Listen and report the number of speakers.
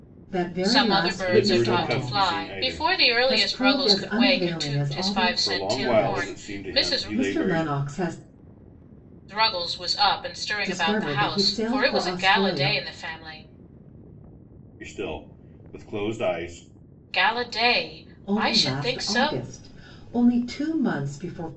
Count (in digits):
3